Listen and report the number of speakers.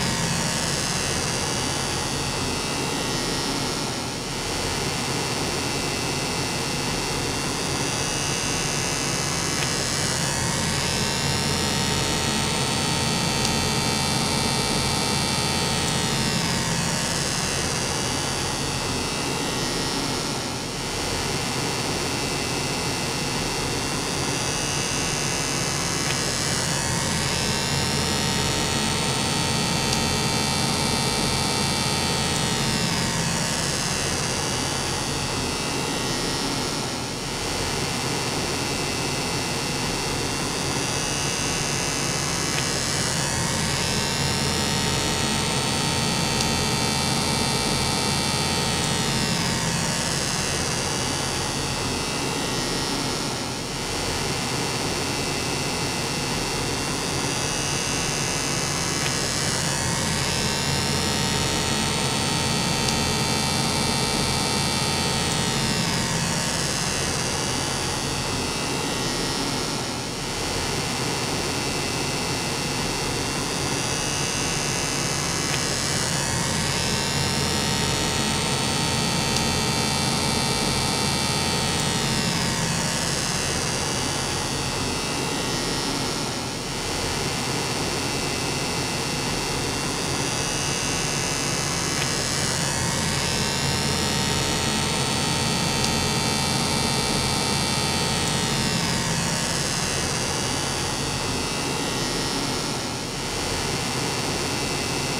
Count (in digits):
0